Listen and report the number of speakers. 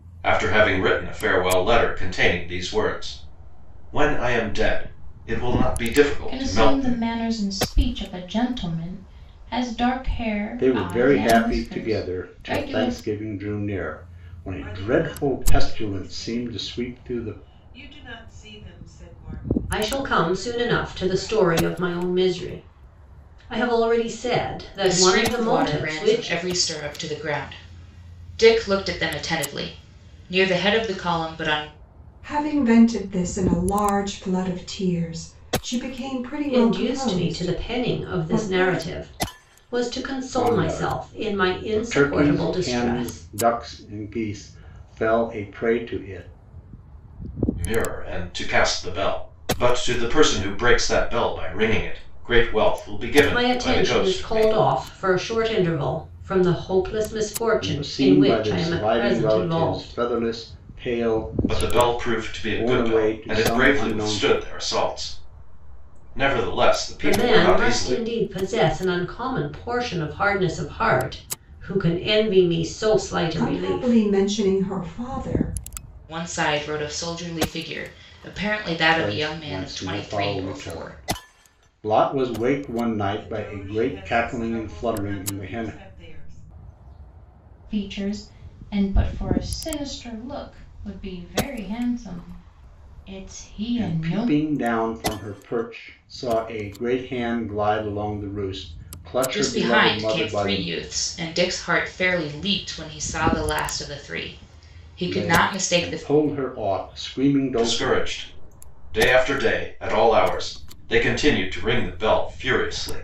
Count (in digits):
7